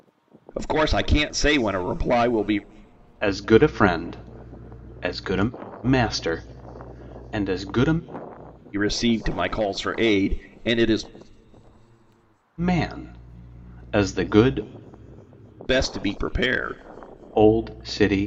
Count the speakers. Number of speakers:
2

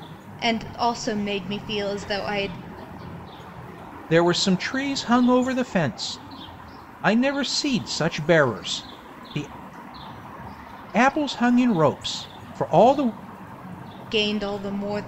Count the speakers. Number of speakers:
2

